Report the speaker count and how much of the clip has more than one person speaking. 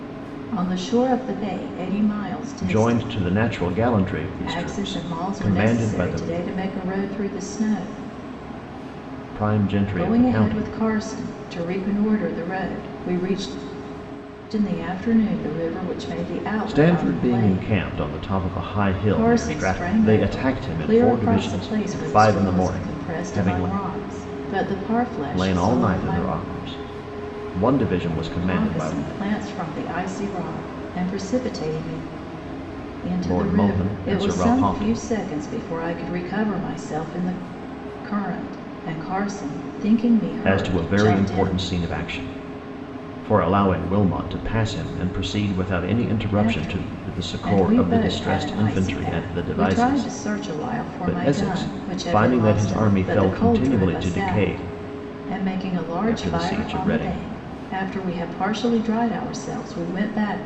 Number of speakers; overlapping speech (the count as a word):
two, about 36%